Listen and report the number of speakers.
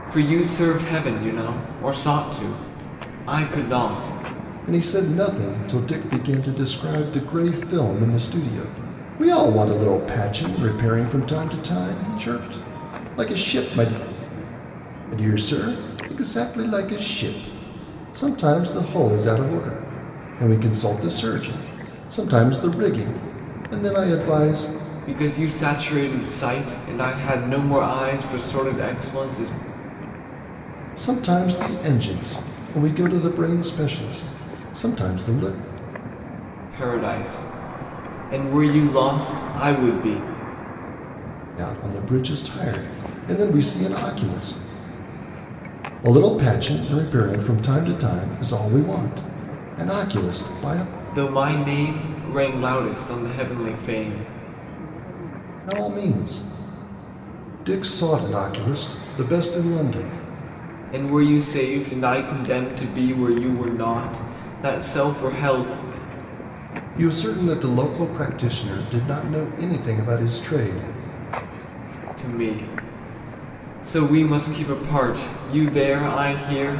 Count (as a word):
two